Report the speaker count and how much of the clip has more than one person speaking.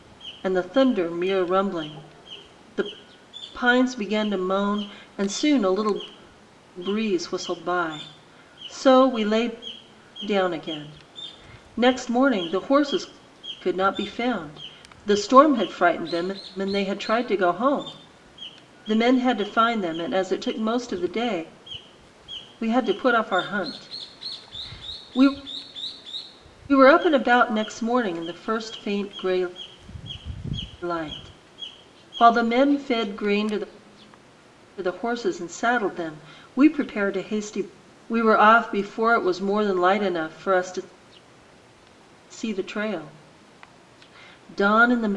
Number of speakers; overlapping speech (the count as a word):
one, no overlap